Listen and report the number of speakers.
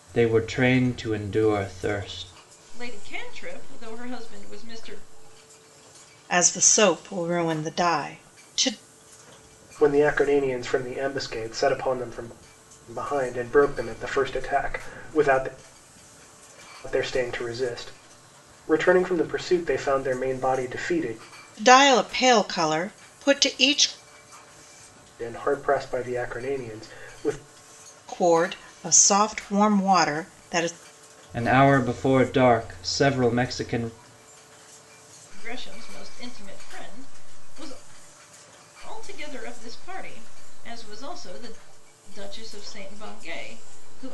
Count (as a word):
four